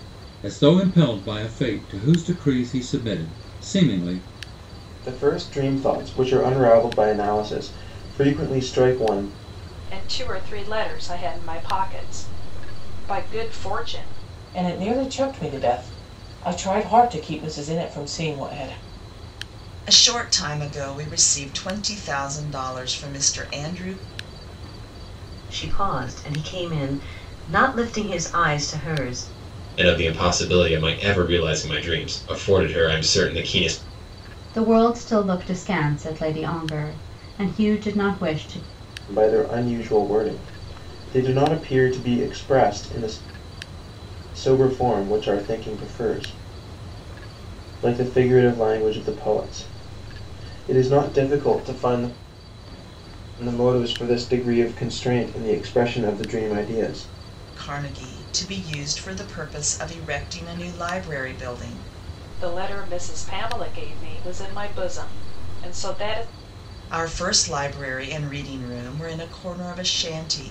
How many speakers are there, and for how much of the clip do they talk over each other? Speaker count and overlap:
8, no overlap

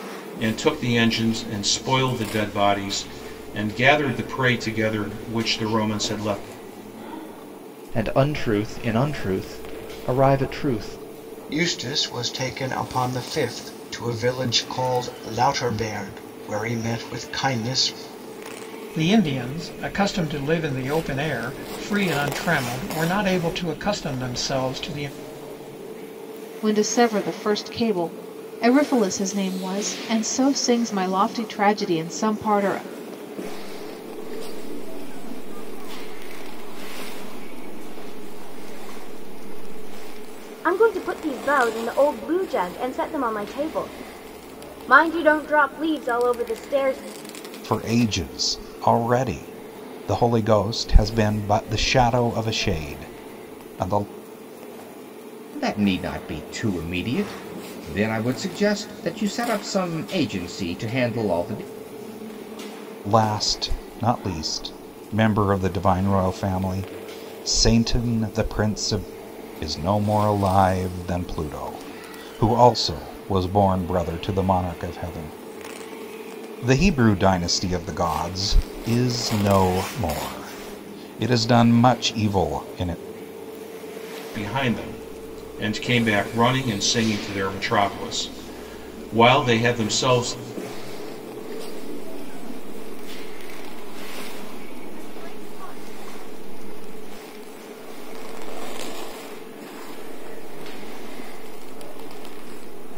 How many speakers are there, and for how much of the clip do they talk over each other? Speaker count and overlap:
9, no overlap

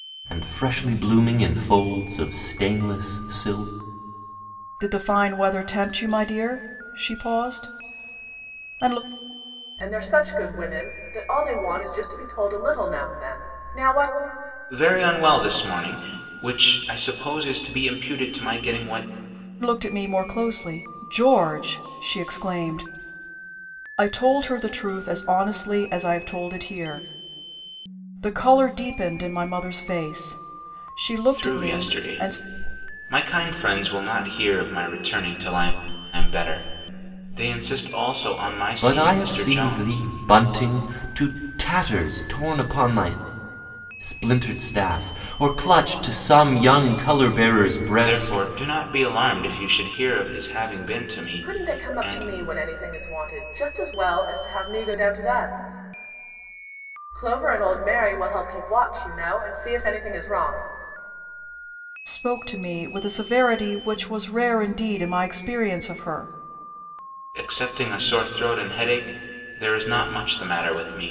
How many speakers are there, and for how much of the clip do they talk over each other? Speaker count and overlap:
4, about 5%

